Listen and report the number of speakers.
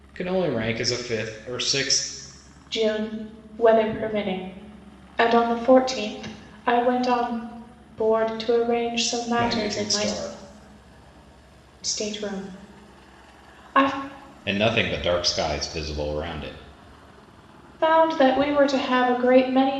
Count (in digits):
2